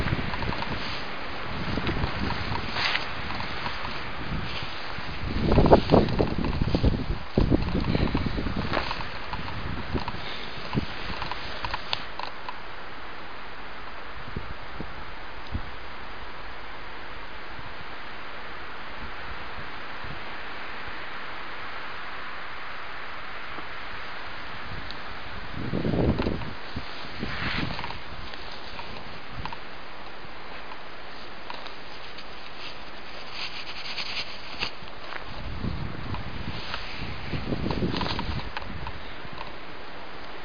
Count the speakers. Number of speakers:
0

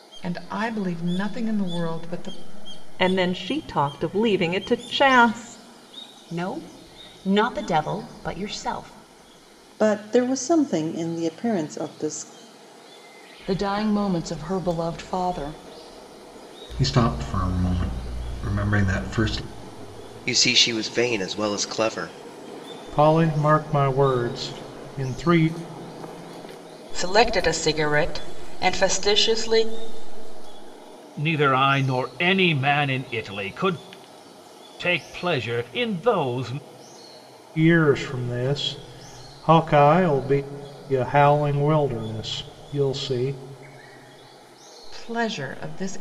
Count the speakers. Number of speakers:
10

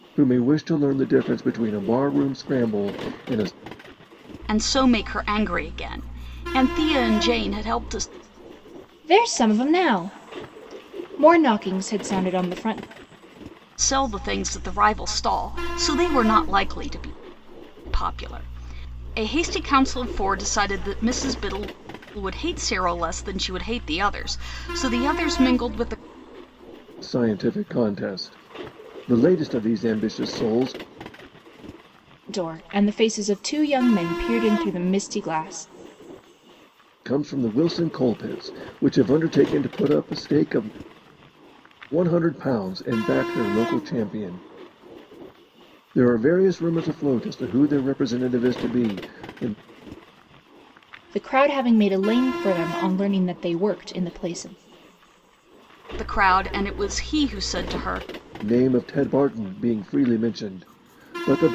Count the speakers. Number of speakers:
3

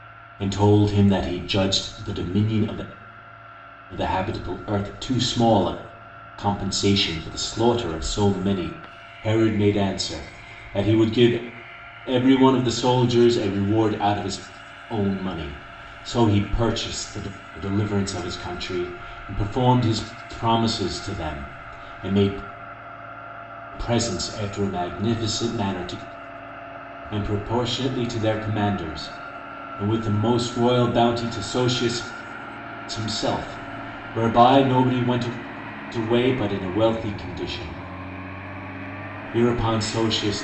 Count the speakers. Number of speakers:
1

